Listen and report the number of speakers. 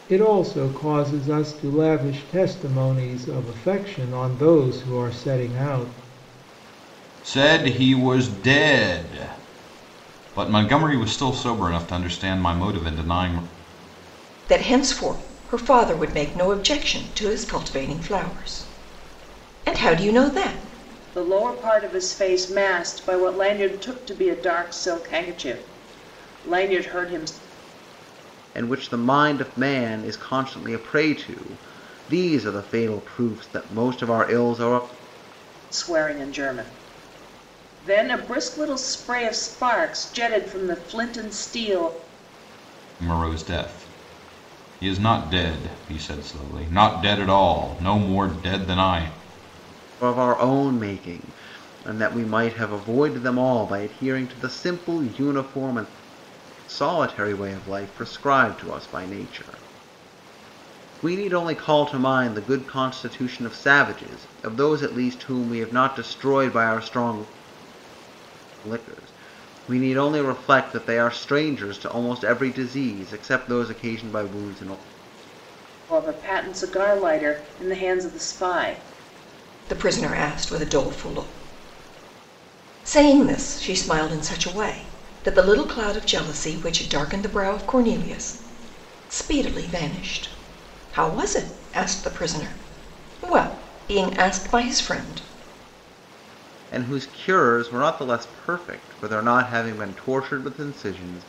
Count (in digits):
5